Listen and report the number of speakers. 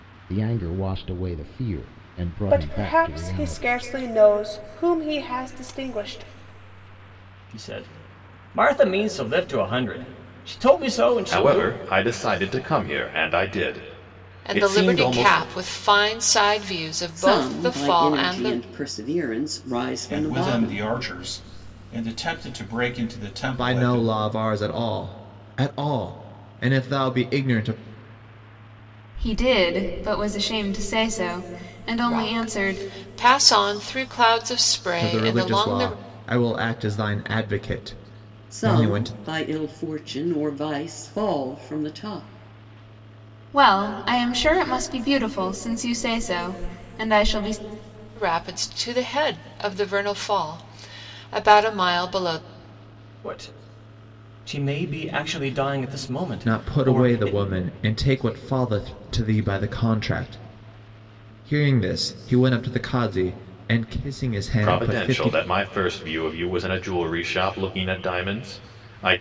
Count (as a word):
nine